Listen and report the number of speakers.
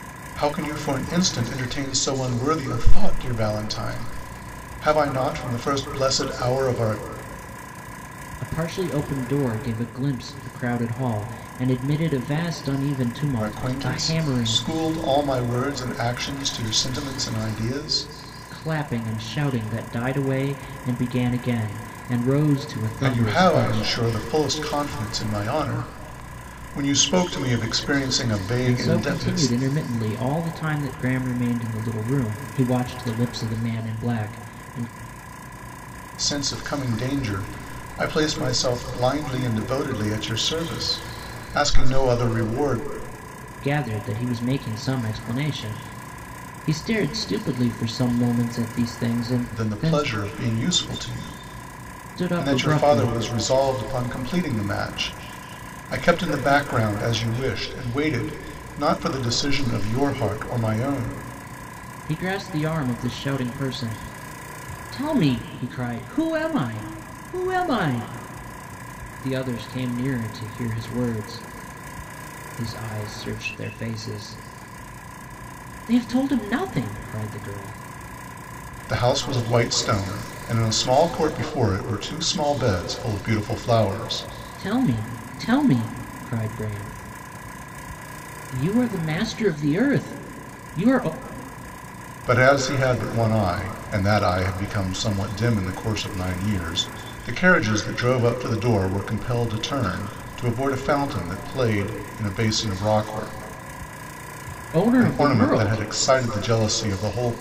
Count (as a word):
two